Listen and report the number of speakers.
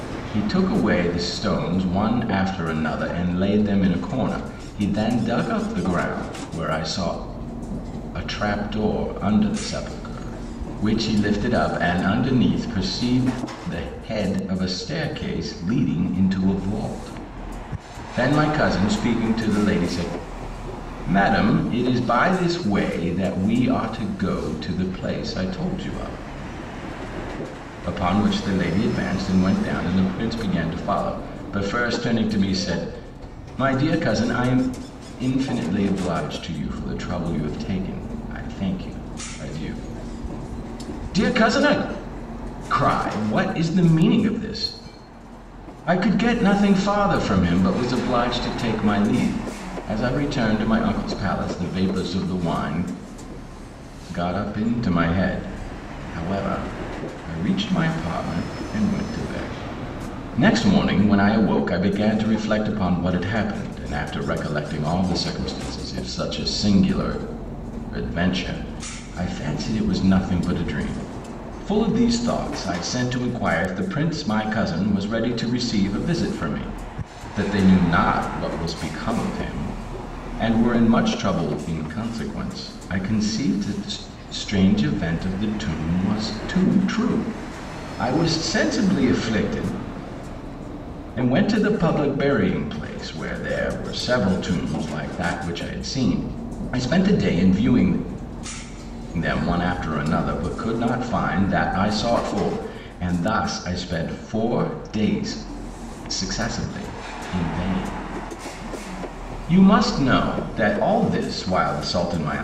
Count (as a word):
one